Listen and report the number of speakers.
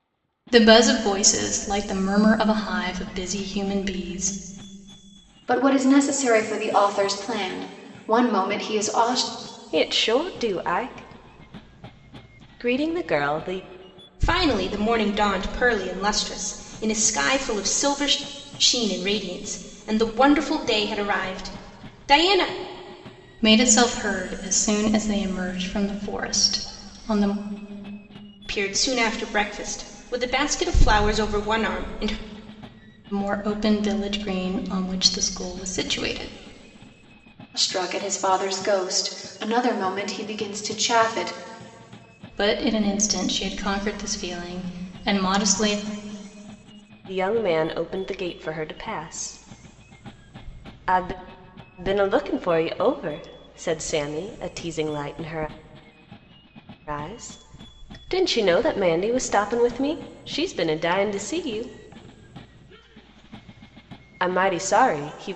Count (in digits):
4